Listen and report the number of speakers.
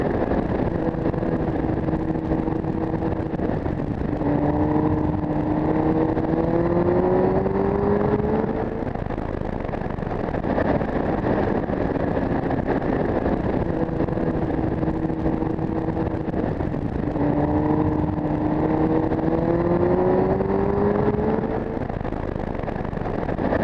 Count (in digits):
0